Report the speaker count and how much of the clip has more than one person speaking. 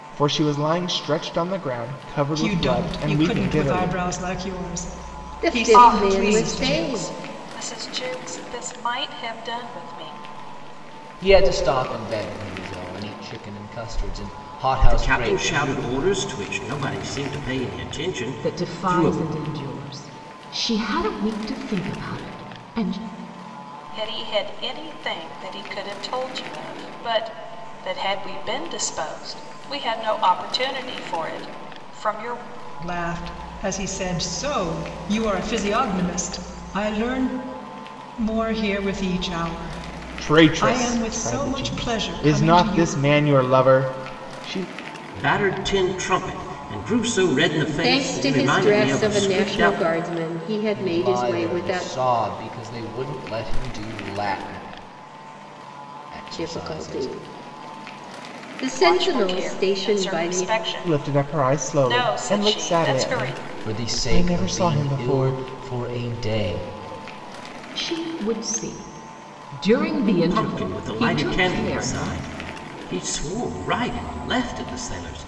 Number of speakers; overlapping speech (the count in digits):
7, about 27%